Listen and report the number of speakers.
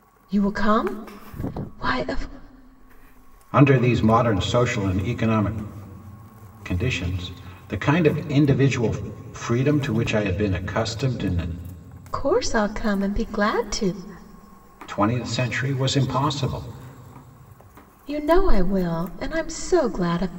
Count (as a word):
two